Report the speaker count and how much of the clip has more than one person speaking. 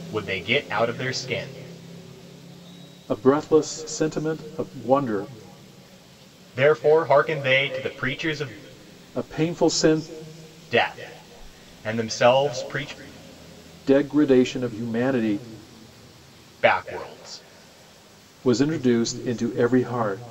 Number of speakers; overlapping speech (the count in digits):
2, no overlap